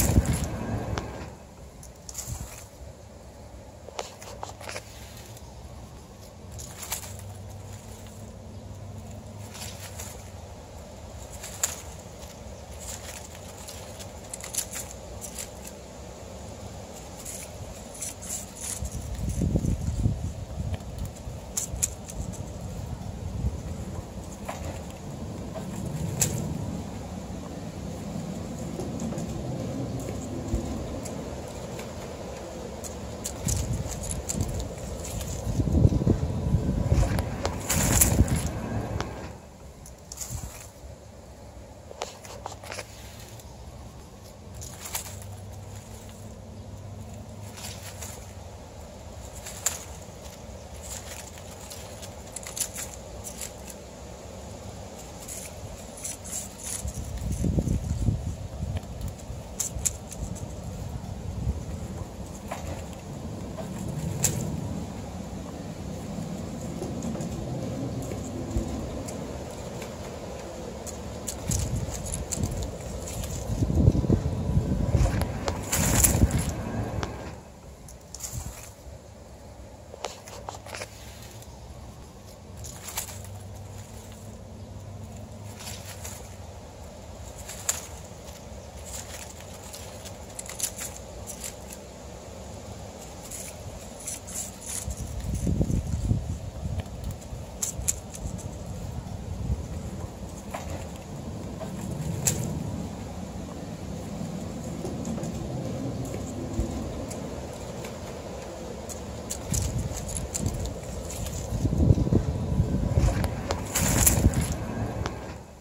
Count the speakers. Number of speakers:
0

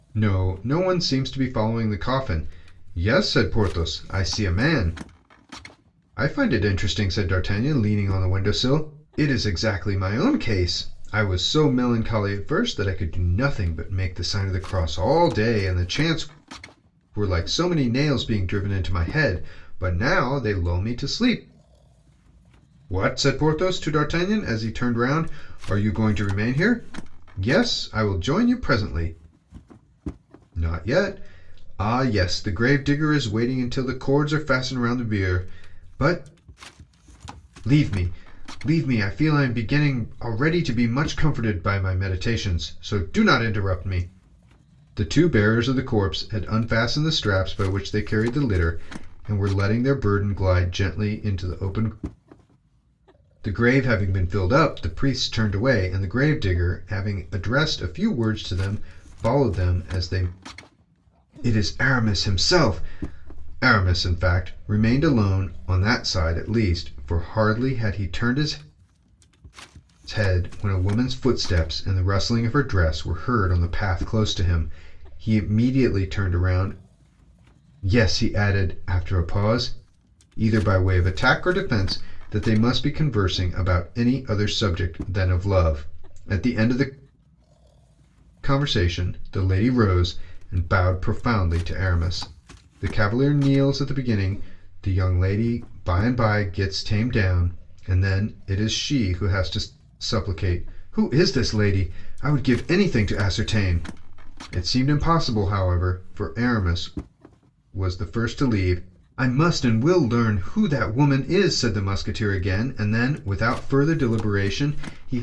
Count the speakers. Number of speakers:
1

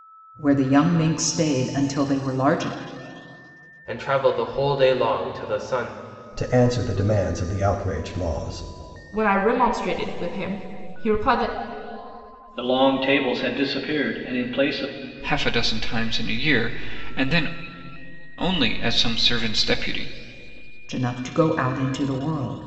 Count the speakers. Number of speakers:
6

